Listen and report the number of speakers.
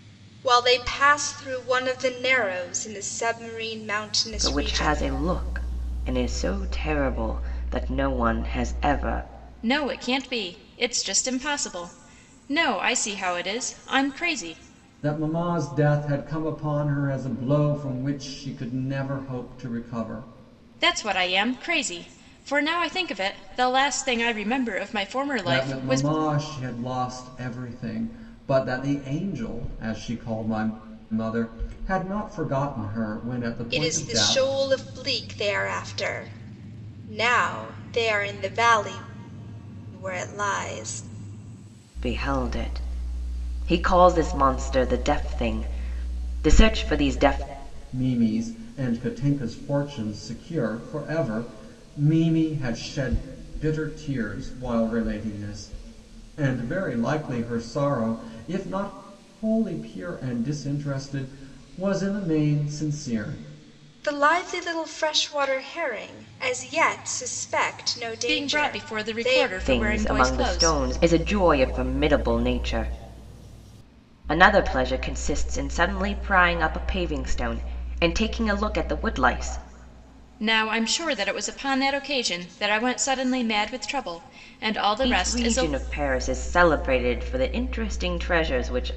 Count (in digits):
4